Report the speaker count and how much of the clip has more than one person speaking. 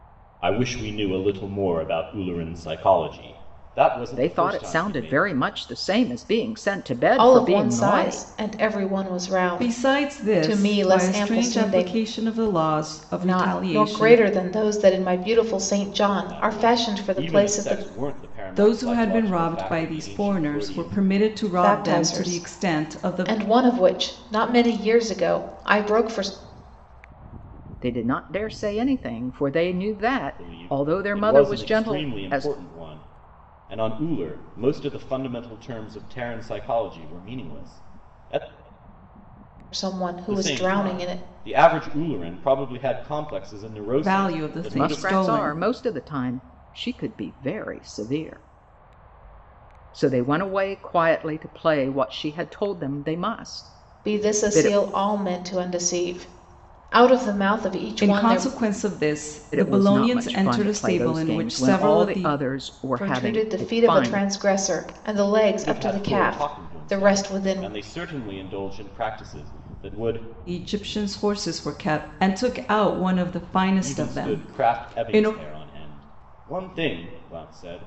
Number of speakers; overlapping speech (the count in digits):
4, about 33%